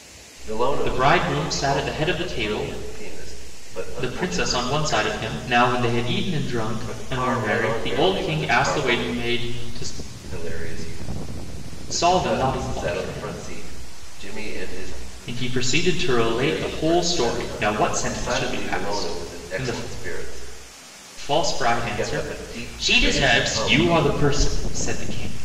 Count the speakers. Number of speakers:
two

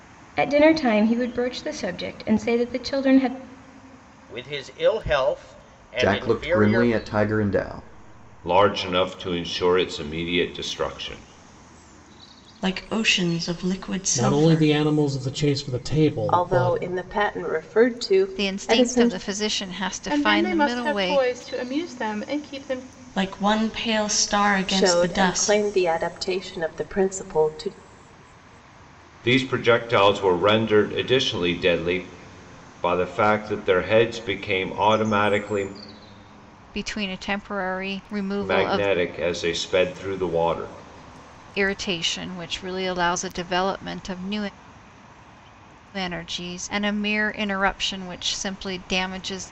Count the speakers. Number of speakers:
nine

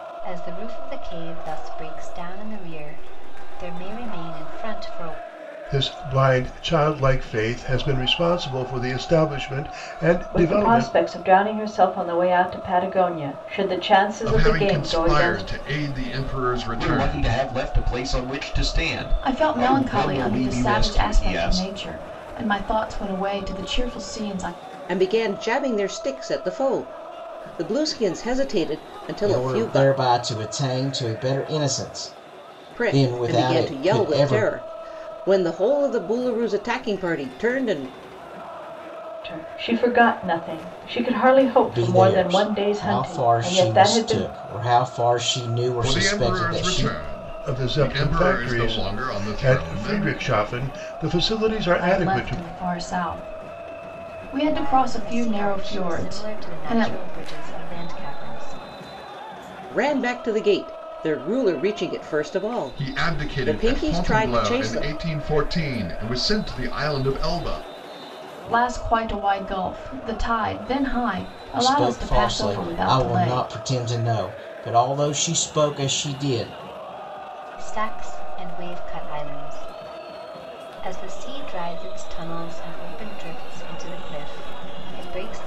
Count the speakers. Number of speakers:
eight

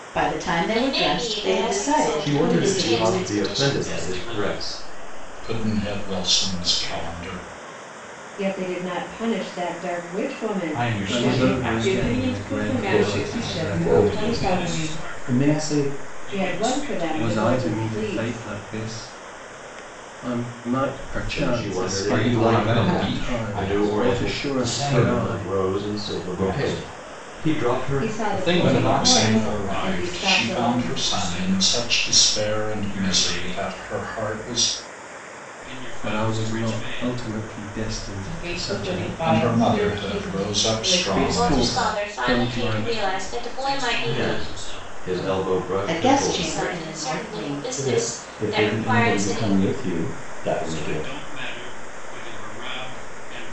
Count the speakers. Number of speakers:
ten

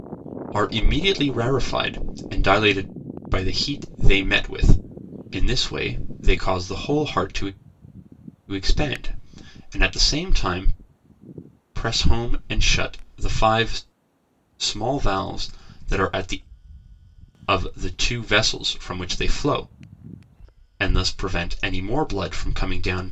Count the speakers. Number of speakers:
one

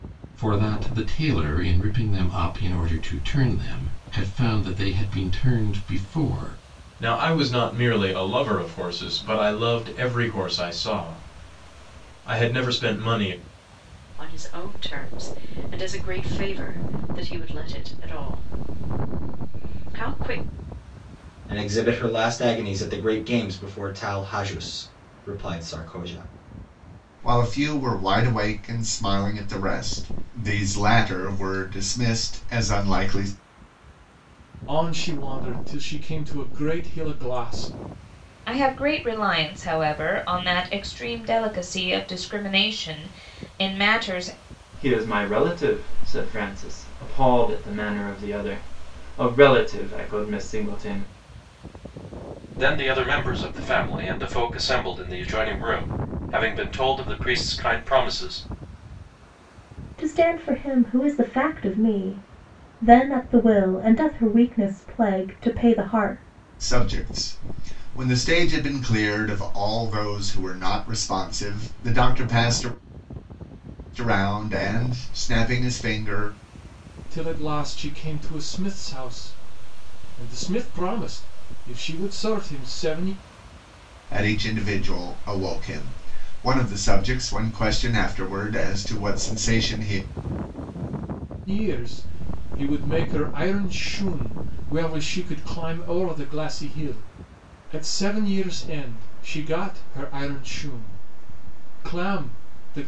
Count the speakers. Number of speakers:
ten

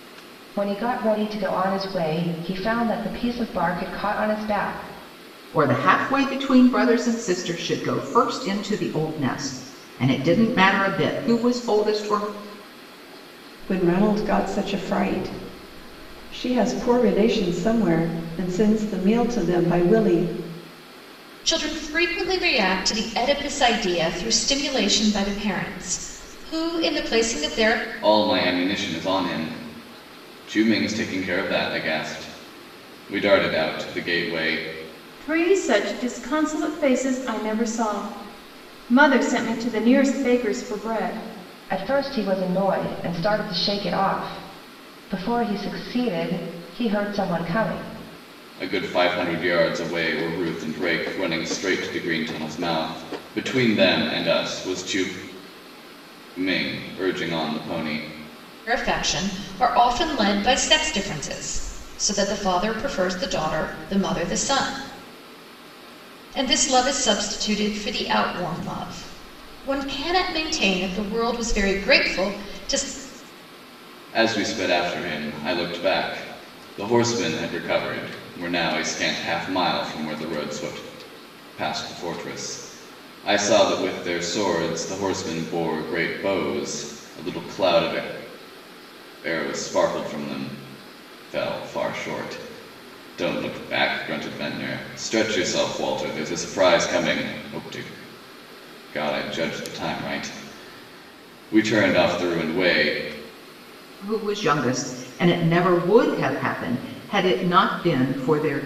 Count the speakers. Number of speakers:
six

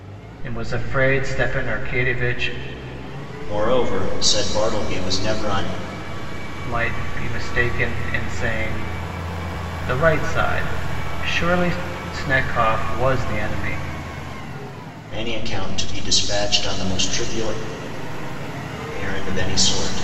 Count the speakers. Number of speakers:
two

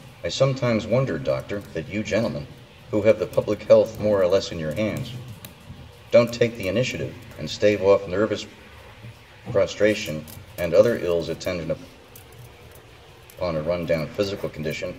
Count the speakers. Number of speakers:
one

